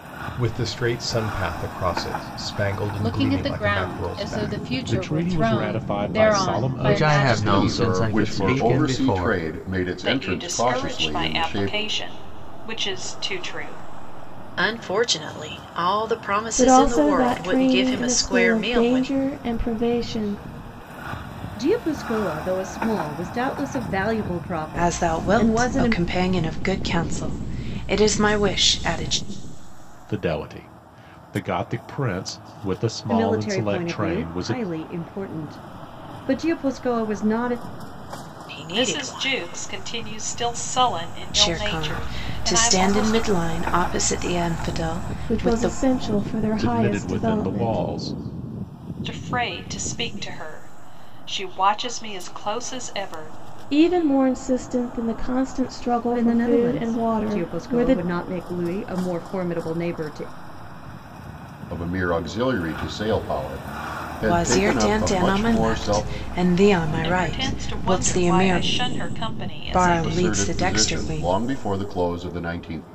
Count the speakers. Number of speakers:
10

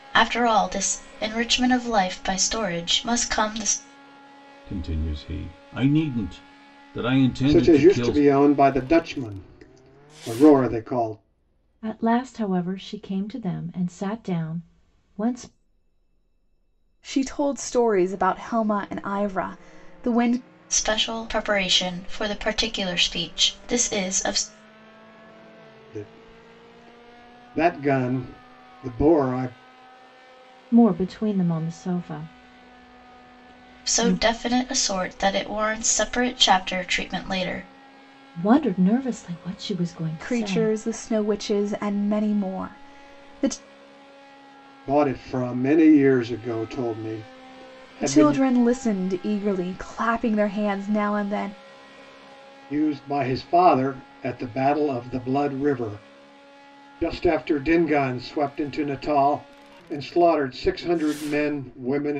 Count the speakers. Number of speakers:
5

